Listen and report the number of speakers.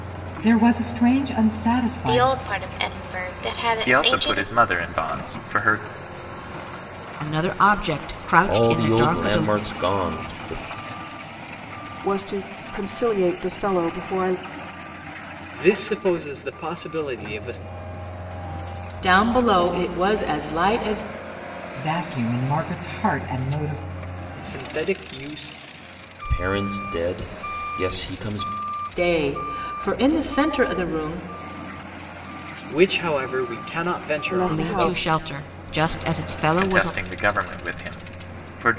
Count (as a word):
eight